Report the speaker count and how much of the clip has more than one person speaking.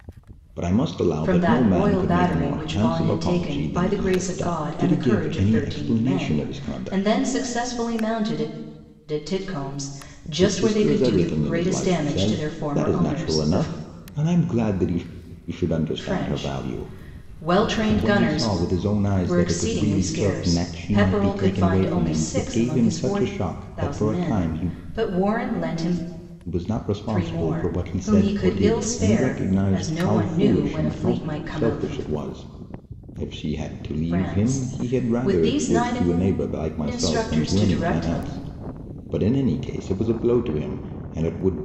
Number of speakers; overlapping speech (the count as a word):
two, about 57%